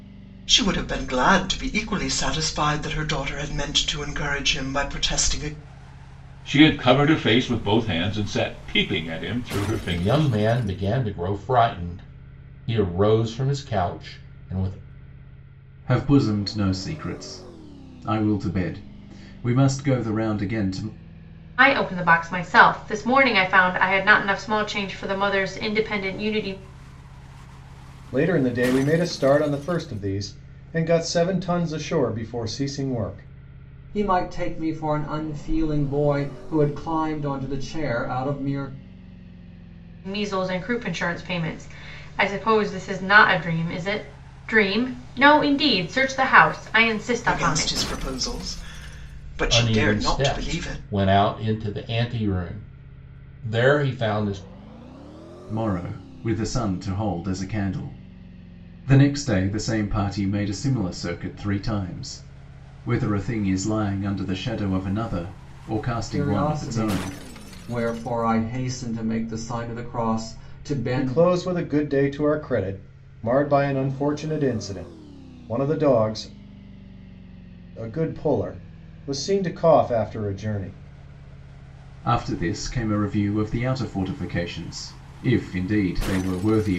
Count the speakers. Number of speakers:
7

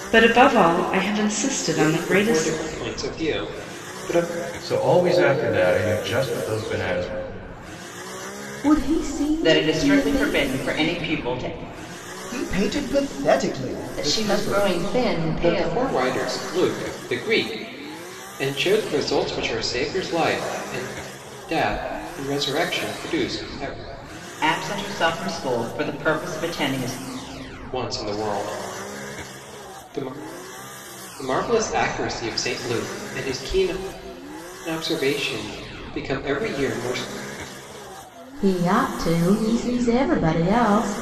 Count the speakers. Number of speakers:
7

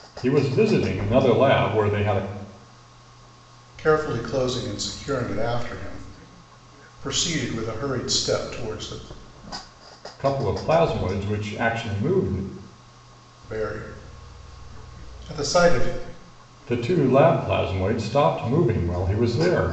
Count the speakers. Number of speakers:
2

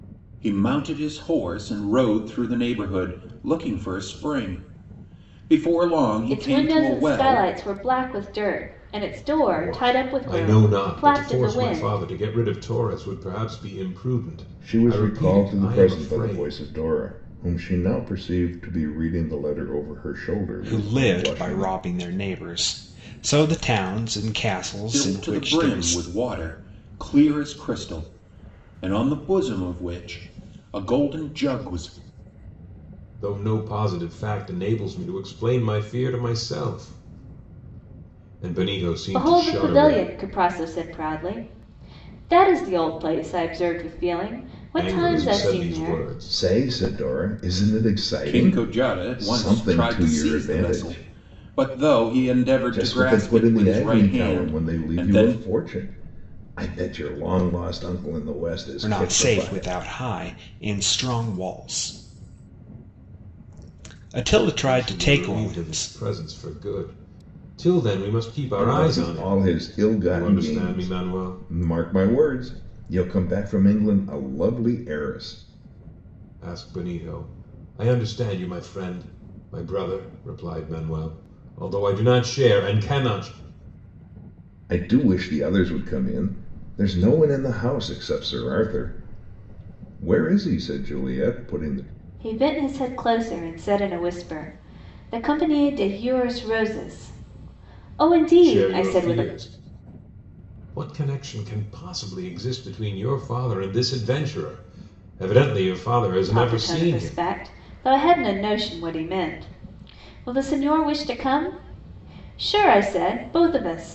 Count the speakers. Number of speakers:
5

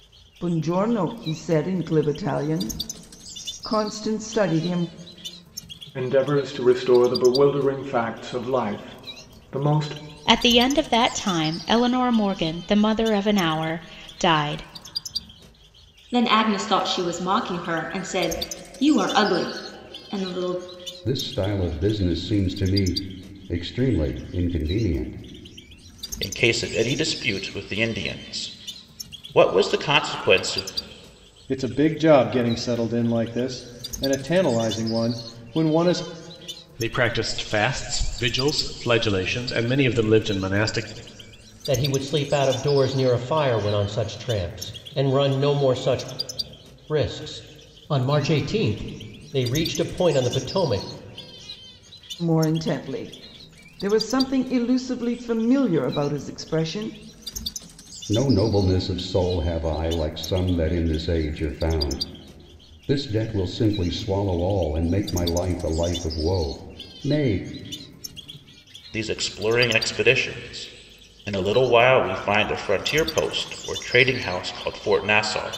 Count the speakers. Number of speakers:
9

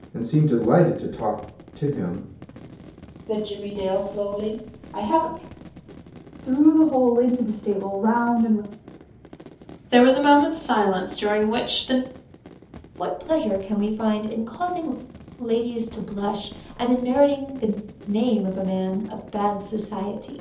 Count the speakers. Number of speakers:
5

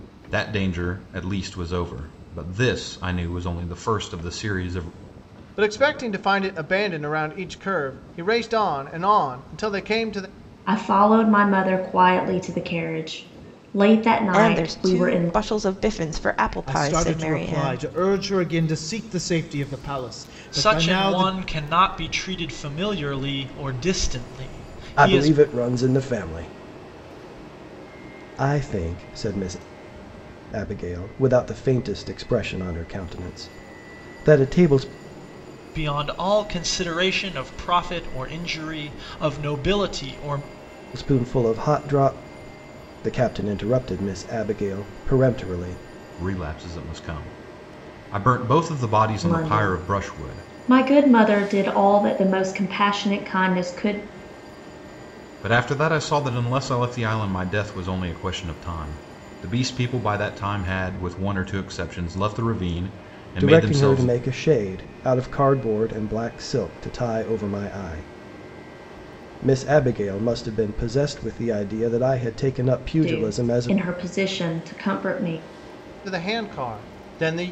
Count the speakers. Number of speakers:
7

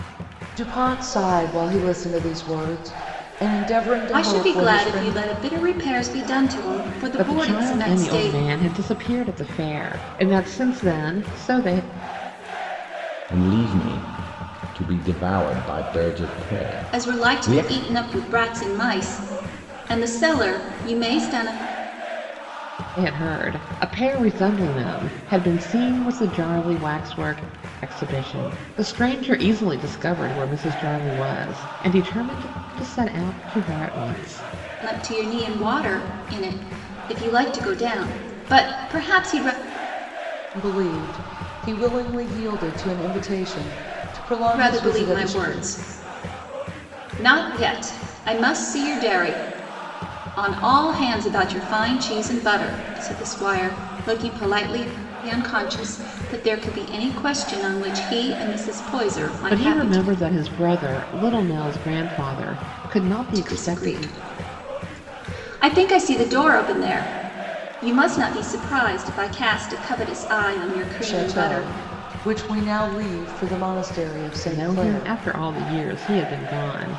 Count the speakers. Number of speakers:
4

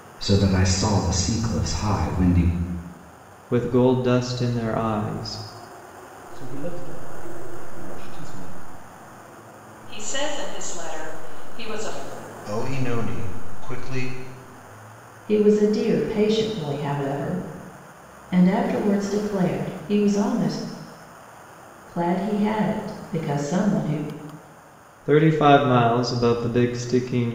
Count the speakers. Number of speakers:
6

